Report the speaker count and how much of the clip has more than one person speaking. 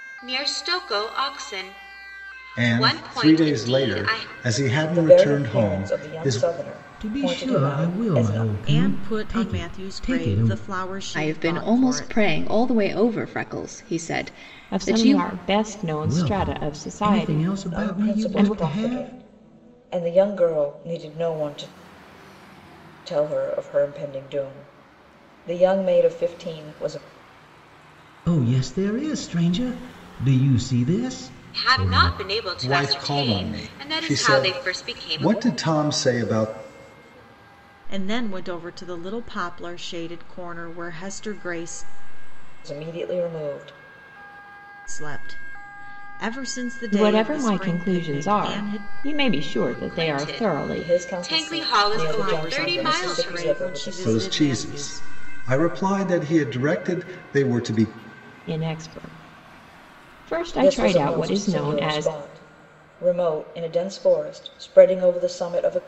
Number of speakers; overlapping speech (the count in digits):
7, about 36%